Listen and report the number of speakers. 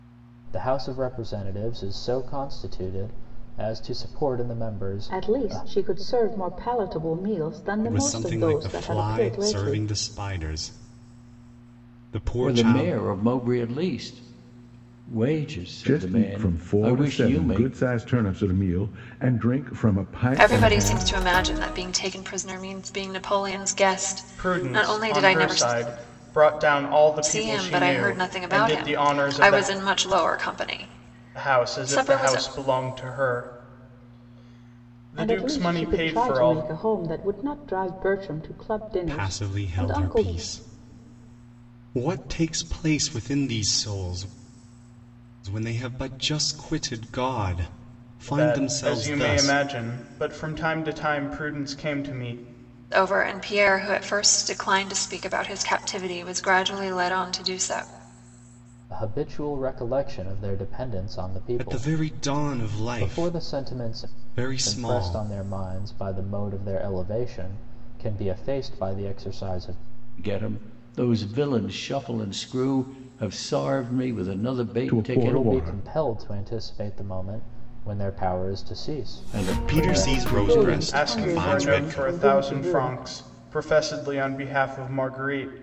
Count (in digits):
7